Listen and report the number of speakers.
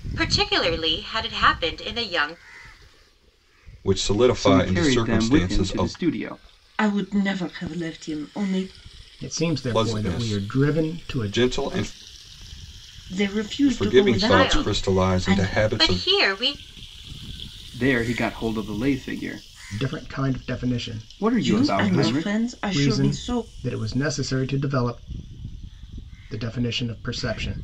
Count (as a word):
five